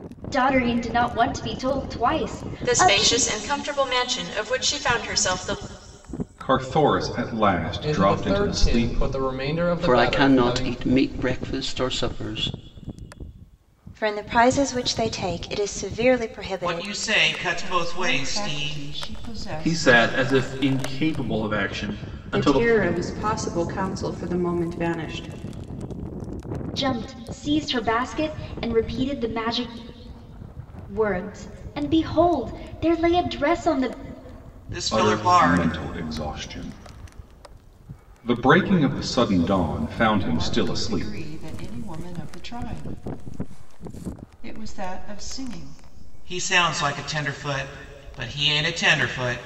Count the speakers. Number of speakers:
ten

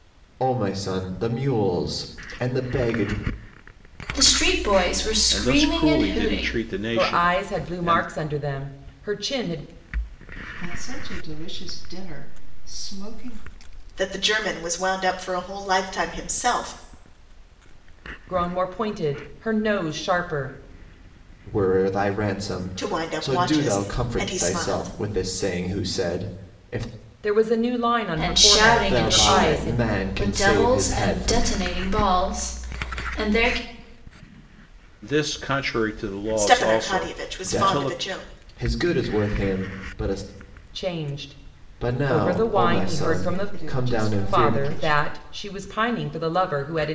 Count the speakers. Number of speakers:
six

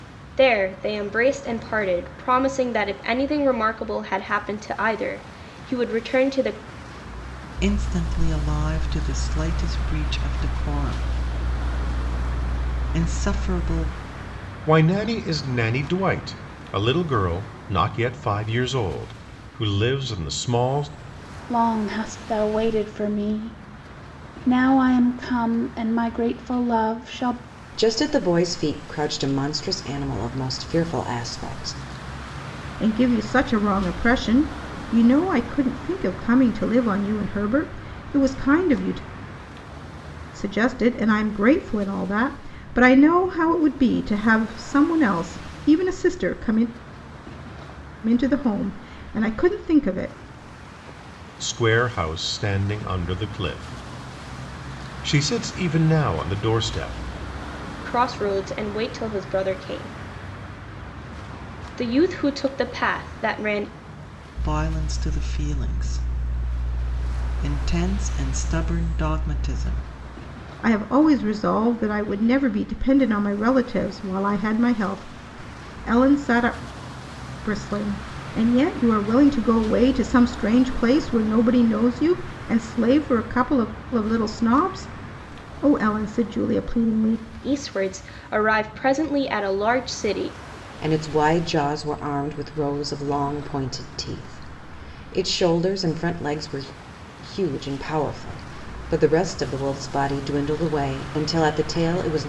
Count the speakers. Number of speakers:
six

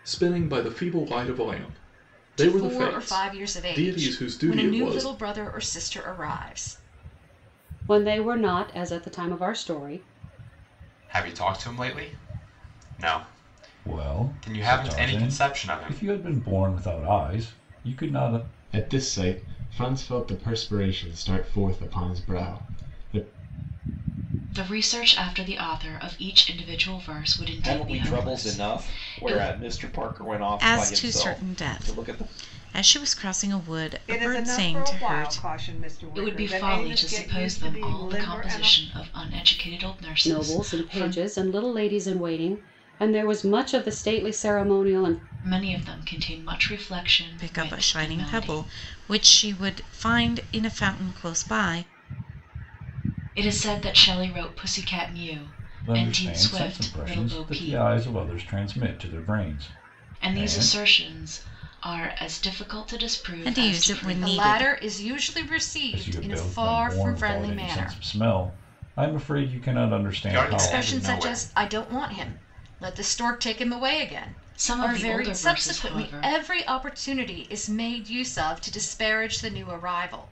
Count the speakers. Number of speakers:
ten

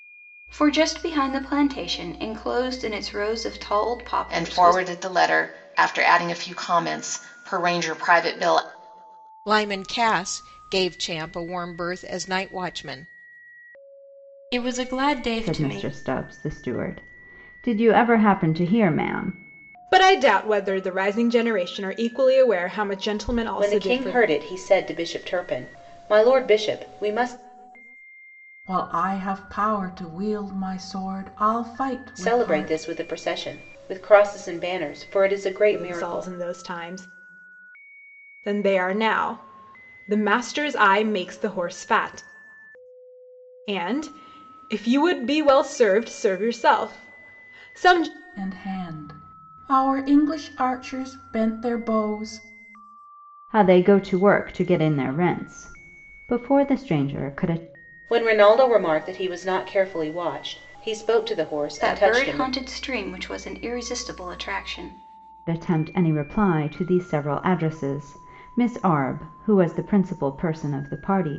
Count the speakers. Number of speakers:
eight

